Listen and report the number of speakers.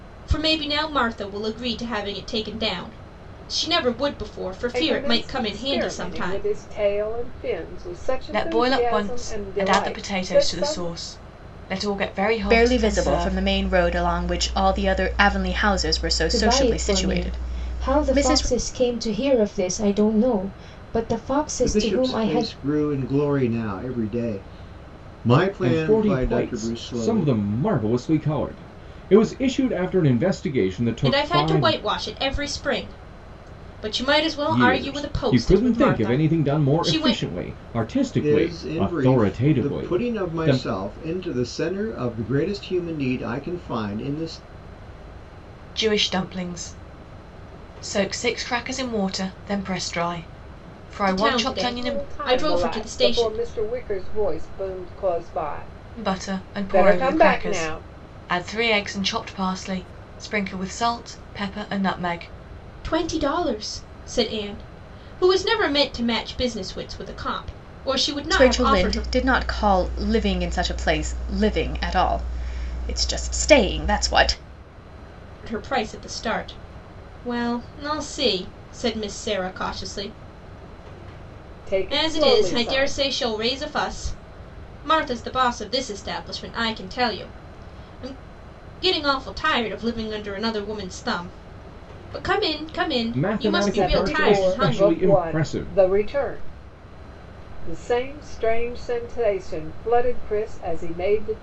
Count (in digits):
7